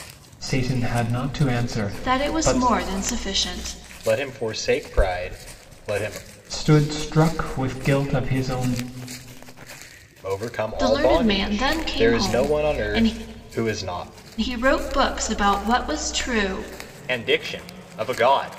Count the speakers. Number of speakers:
3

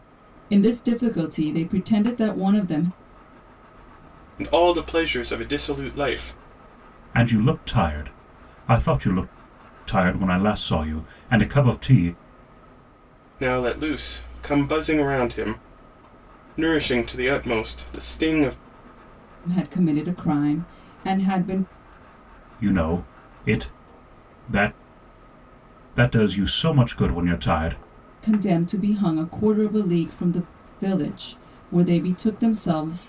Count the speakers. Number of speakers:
3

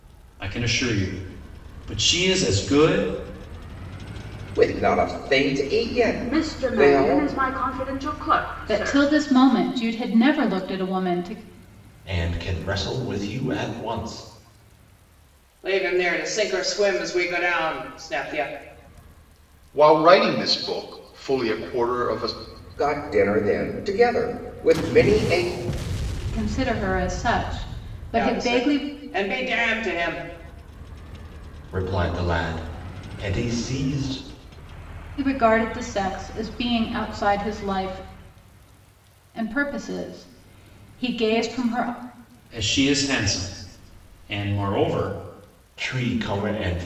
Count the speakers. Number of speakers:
7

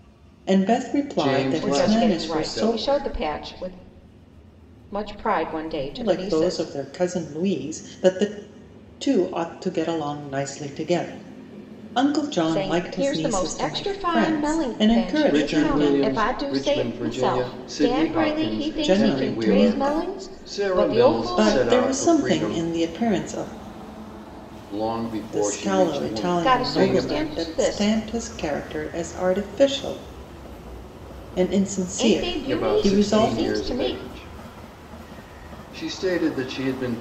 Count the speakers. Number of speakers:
3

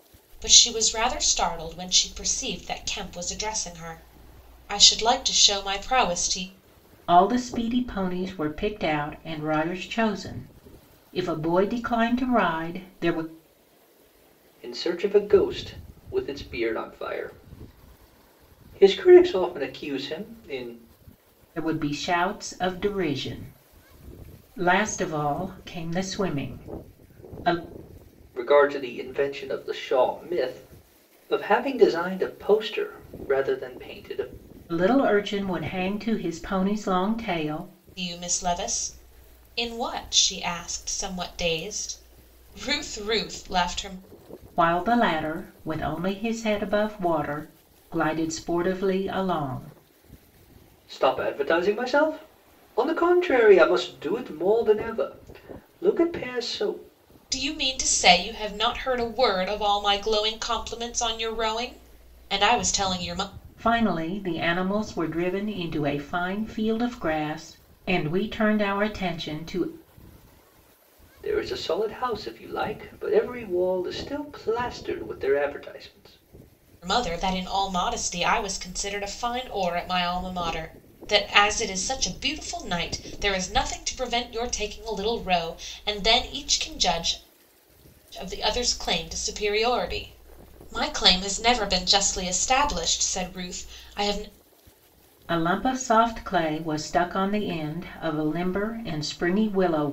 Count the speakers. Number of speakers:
3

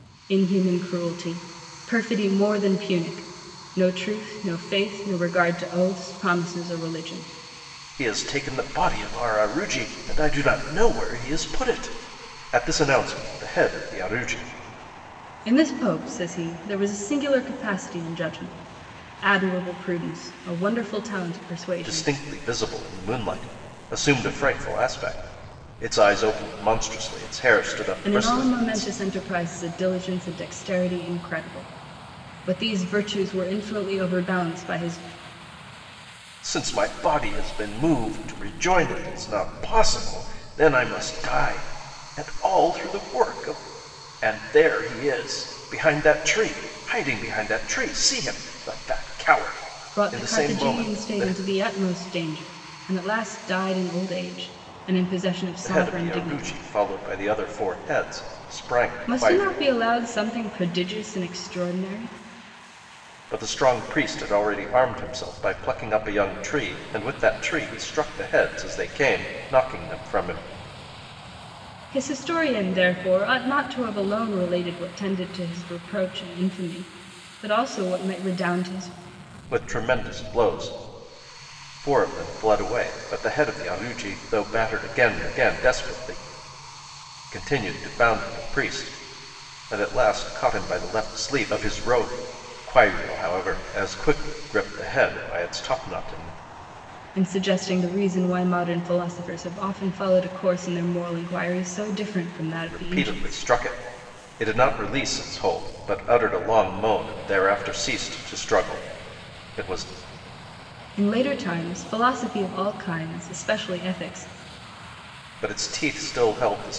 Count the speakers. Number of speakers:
2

